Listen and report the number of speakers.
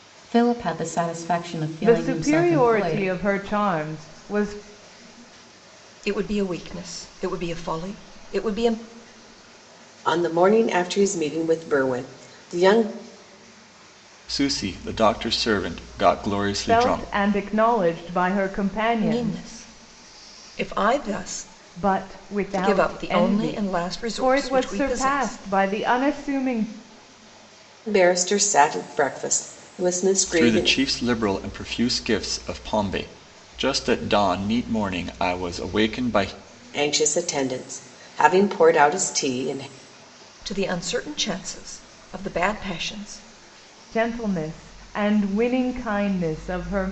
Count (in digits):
5